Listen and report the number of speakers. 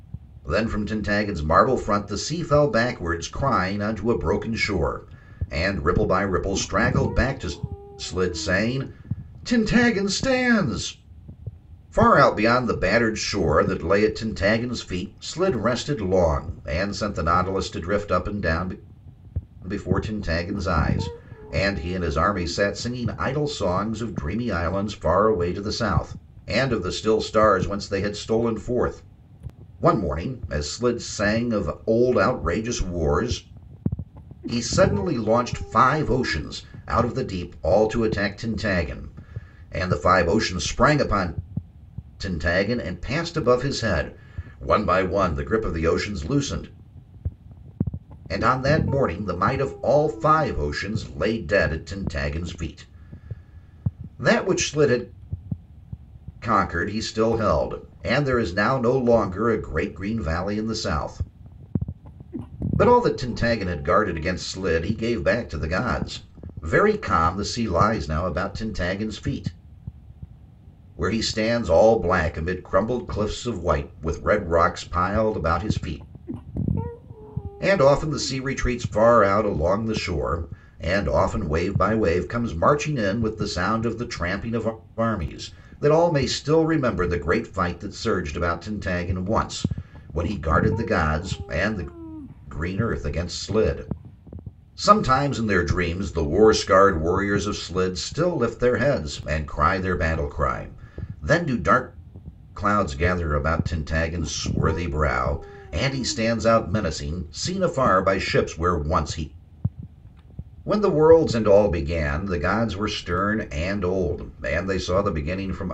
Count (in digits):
1